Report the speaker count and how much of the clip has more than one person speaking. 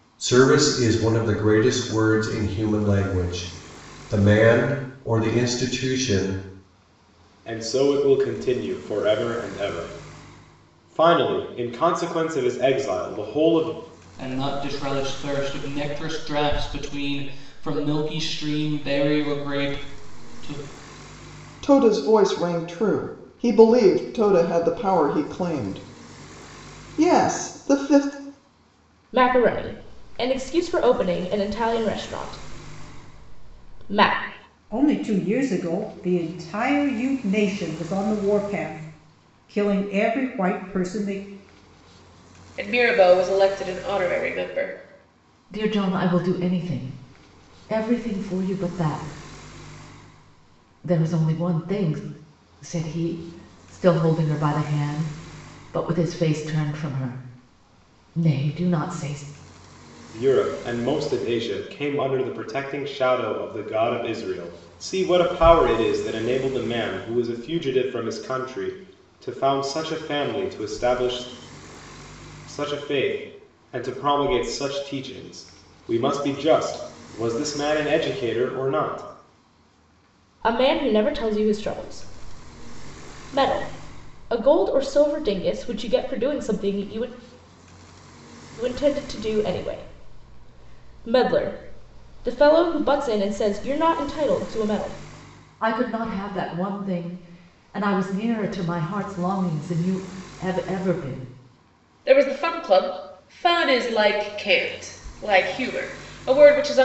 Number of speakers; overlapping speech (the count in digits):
8, no overlap